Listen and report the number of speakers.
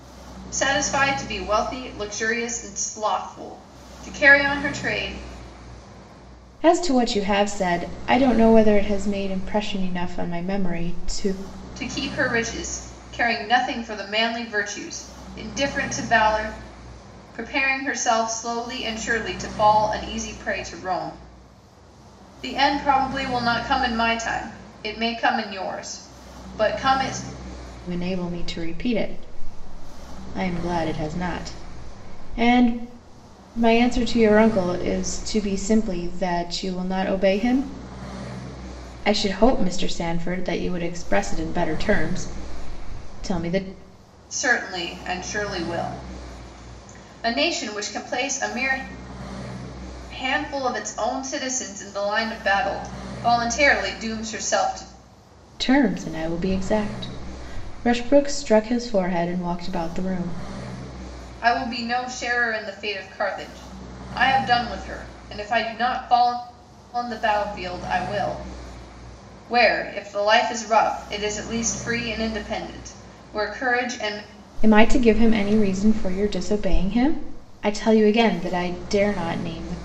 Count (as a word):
two